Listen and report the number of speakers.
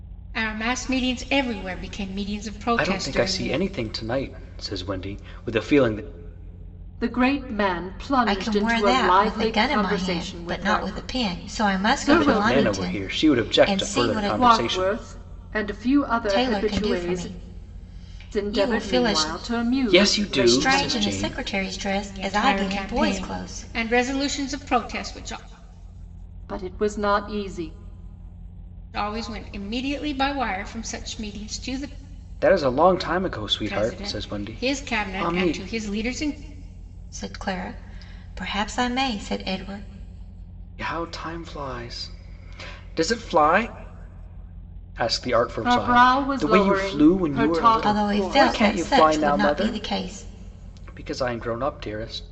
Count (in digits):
4